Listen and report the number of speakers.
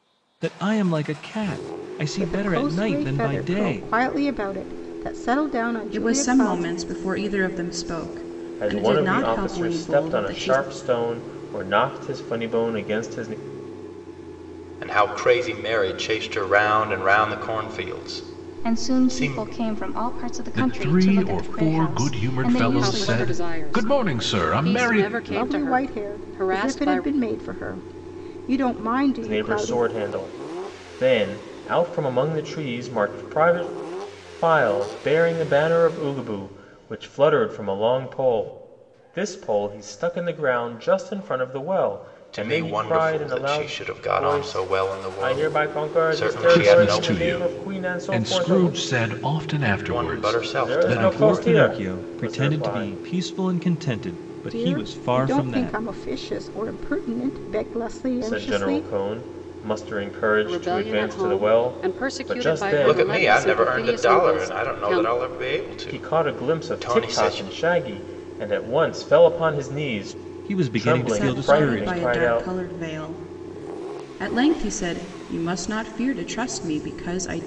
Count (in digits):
8